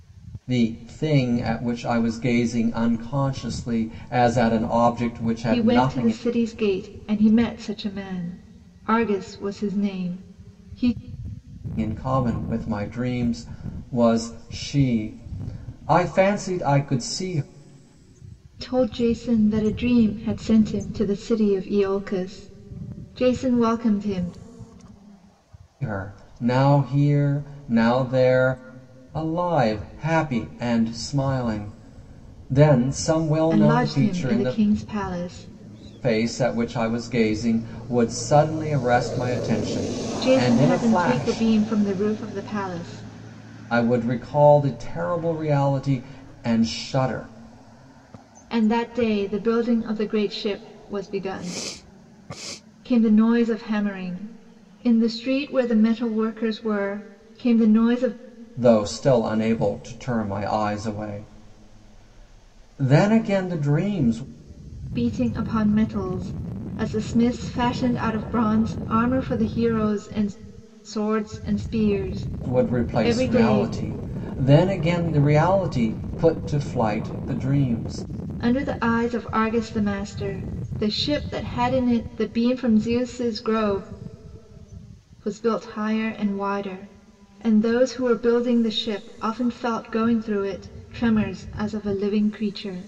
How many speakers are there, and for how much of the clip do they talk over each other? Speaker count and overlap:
2, about 5%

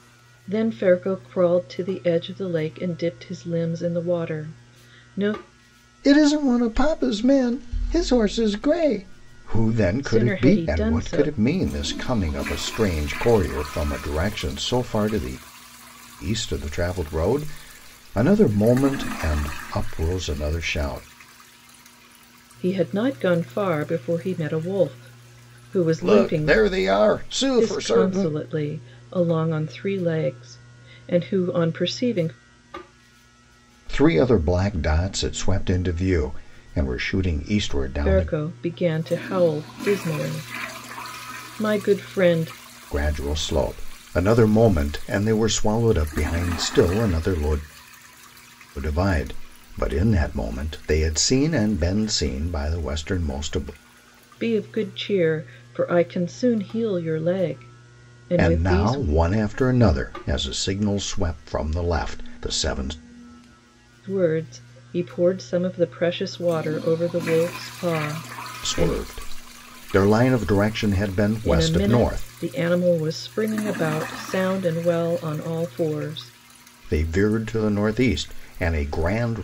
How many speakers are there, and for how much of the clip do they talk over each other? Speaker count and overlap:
2, about 6%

